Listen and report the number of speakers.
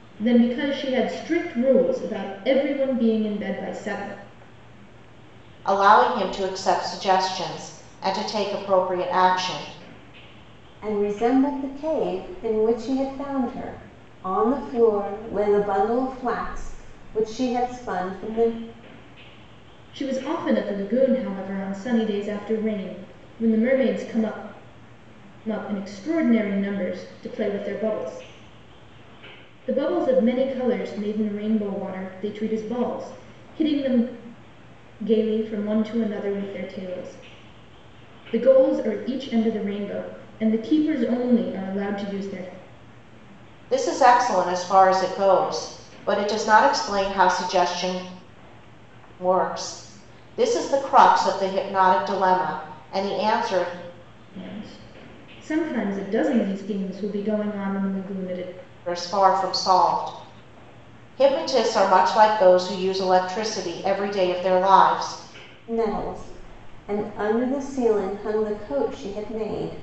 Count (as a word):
three